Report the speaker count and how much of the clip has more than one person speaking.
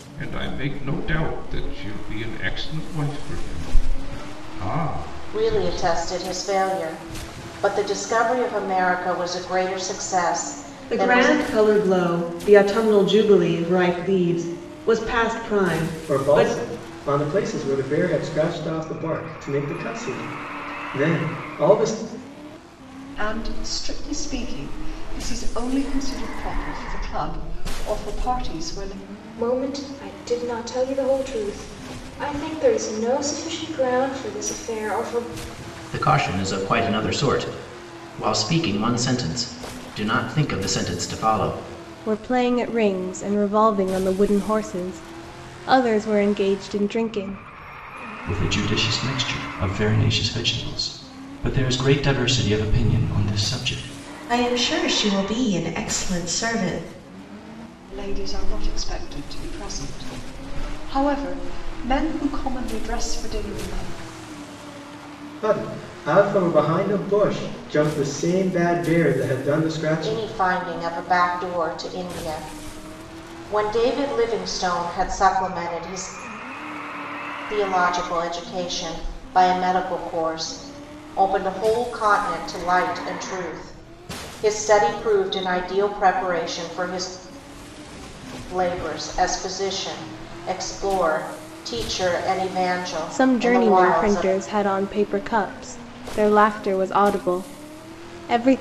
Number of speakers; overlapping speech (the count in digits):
10, about 3%